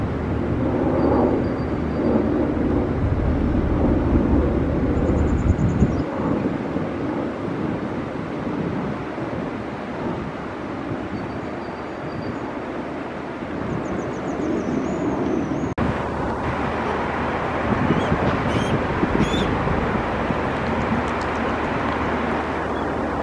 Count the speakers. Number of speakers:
0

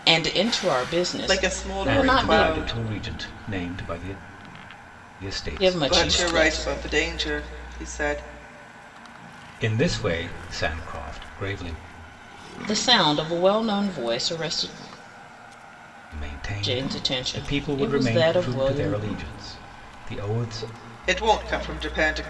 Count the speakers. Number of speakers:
3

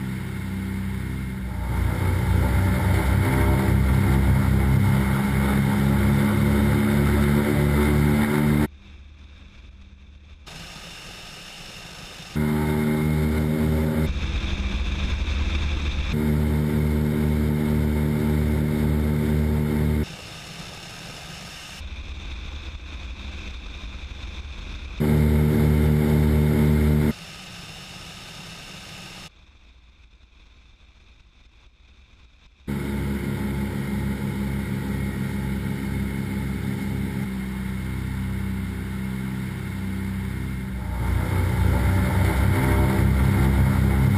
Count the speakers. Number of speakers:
0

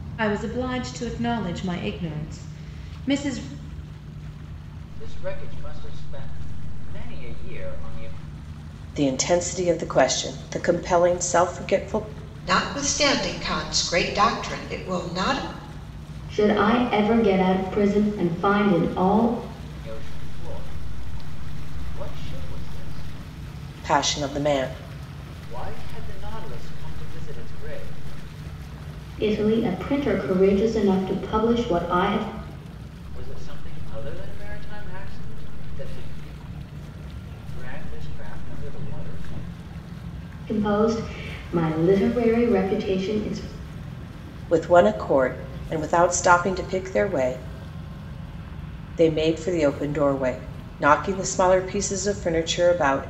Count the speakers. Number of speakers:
5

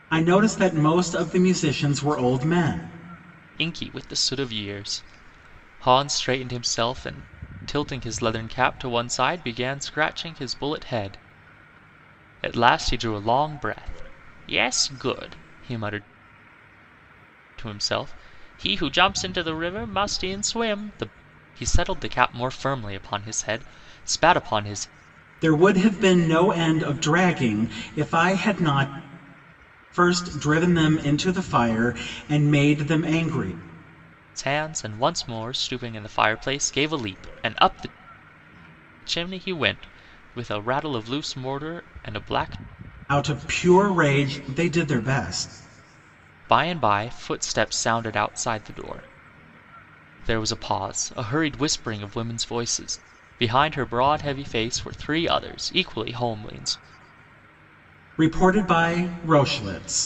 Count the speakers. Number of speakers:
2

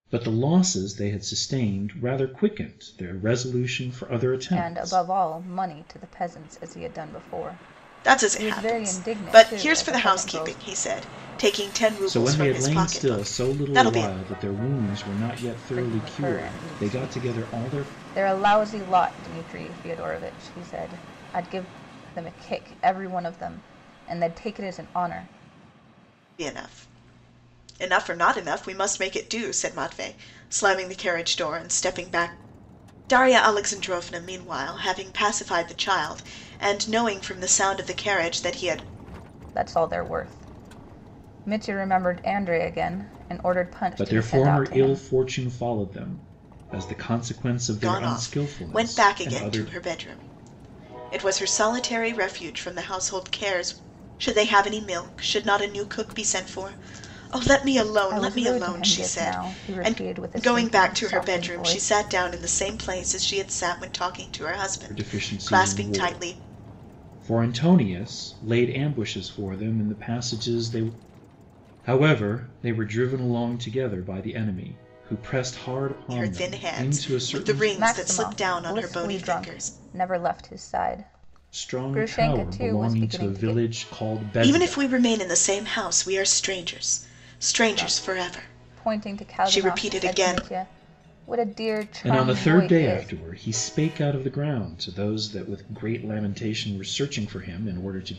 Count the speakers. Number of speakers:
3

